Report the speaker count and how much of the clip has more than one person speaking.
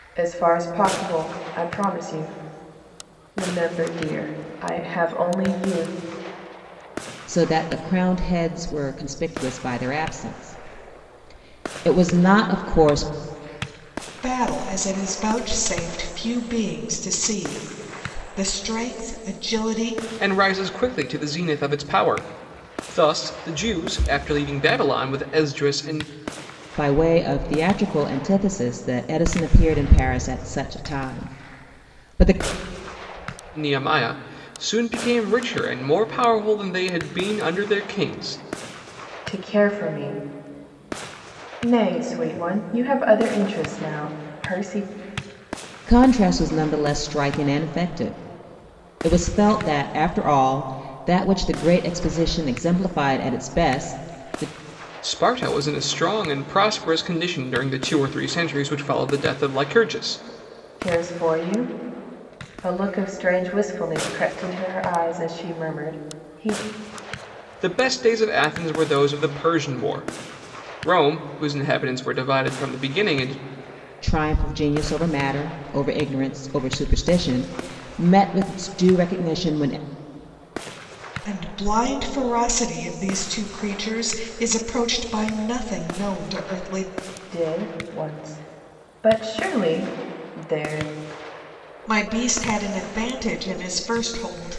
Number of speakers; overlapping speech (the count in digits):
4, no overlap